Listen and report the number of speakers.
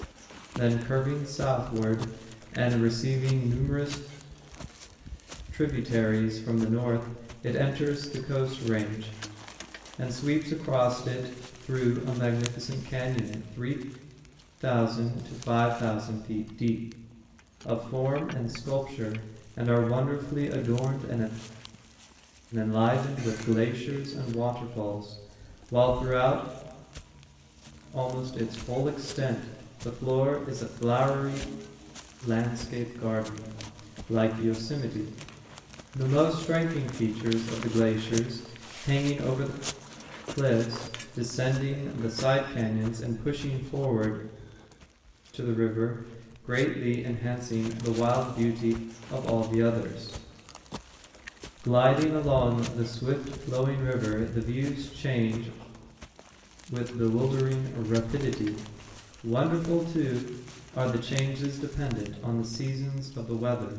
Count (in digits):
1